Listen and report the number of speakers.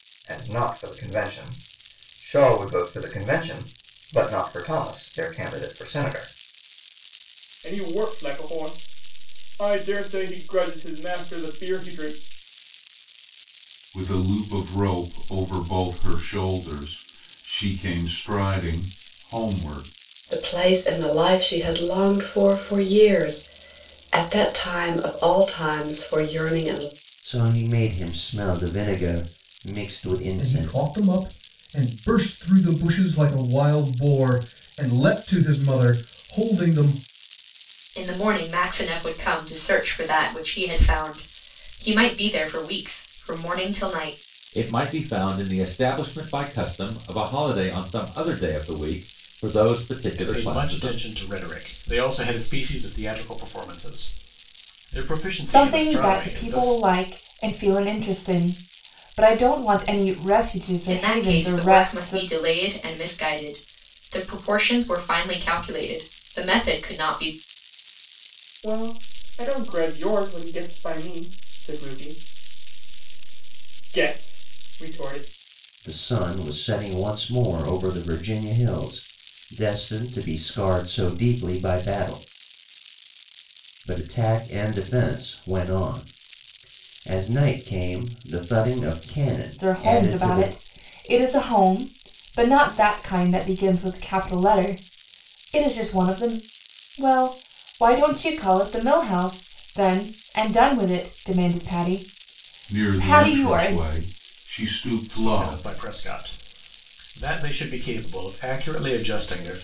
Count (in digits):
10